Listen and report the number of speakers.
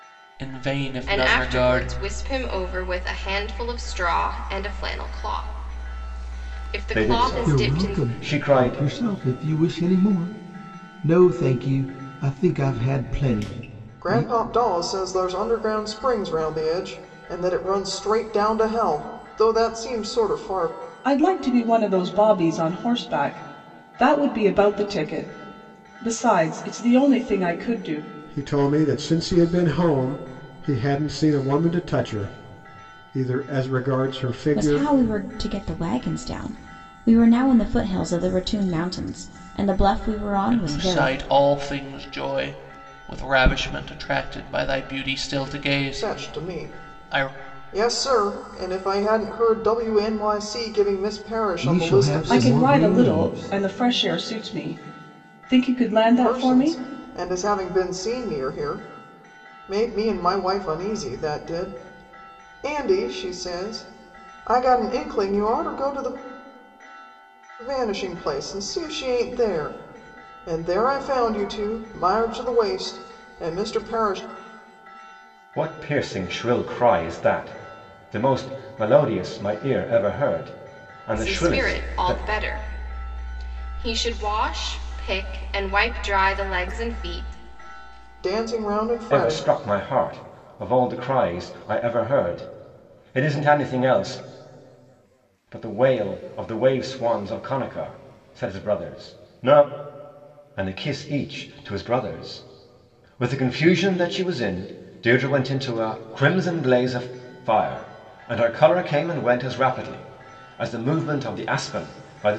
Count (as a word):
eight